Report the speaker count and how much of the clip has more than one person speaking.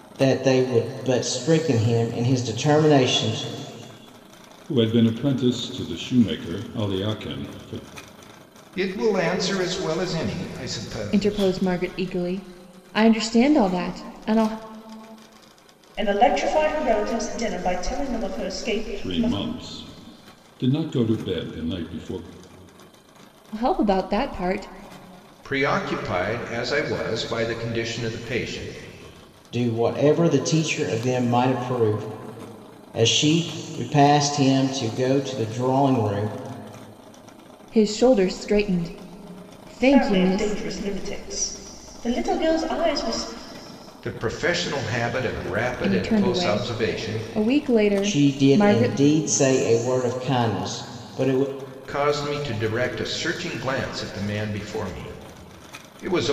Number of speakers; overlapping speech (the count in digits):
5, about 8%